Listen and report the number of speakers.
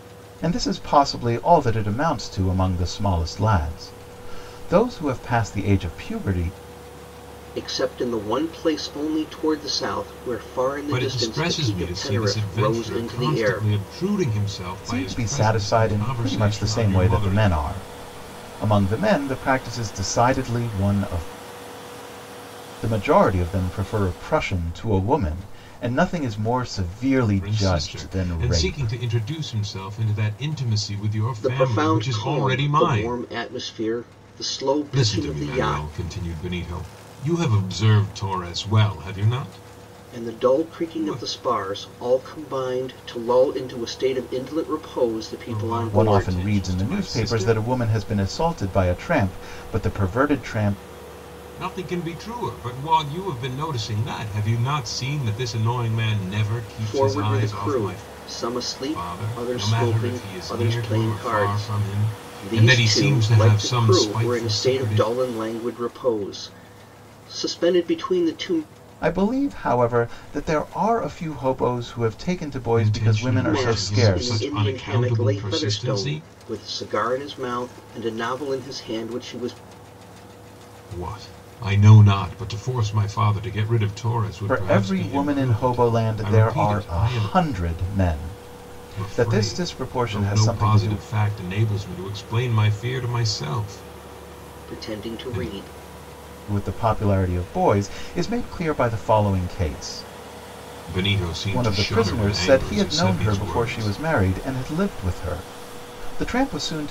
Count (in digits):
3